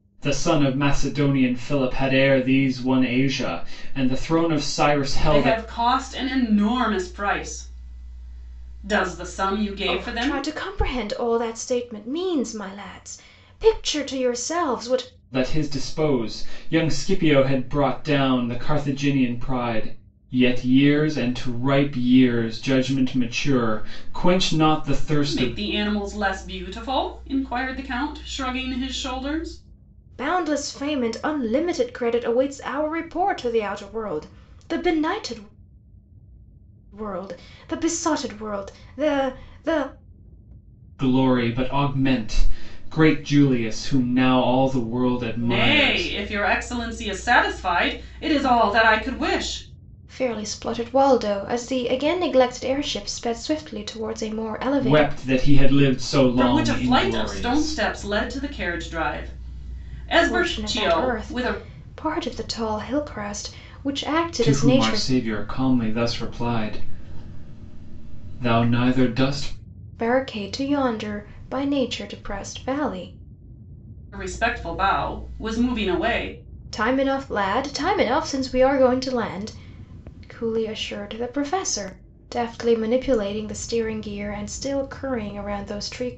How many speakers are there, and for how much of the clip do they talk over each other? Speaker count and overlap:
three, about 7%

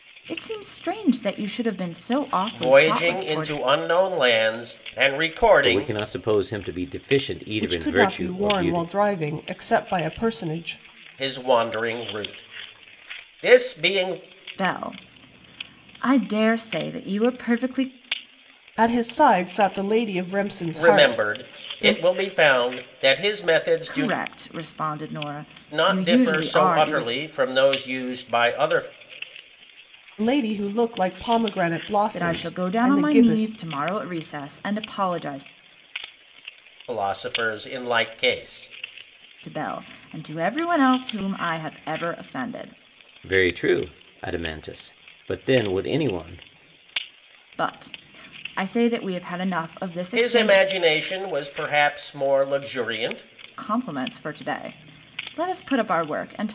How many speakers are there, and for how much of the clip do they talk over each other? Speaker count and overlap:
four, about 14%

